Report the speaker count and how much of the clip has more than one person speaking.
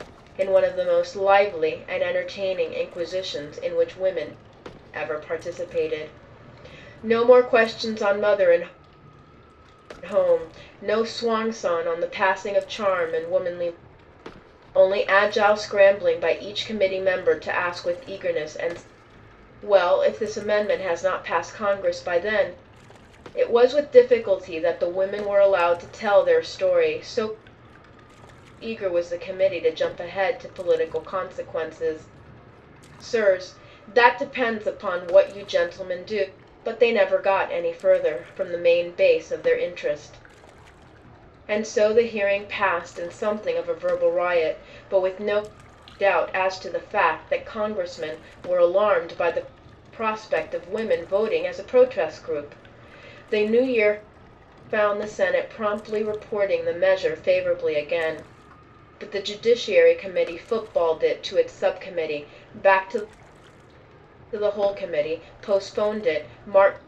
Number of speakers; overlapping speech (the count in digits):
1, no overlap